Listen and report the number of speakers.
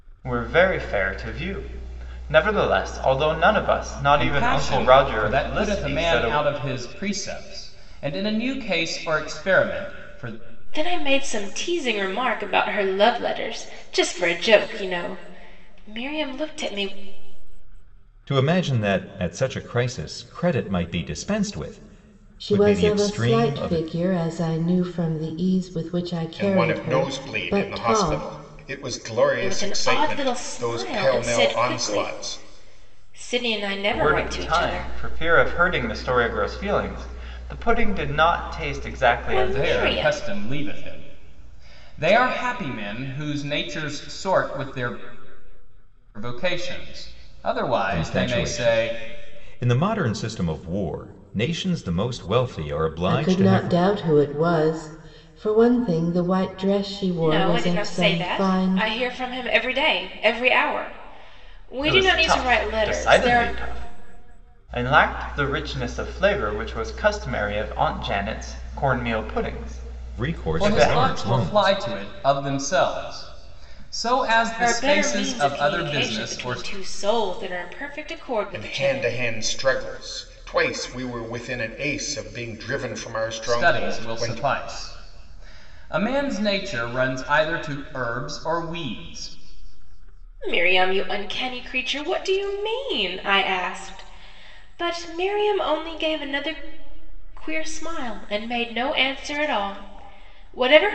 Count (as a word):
six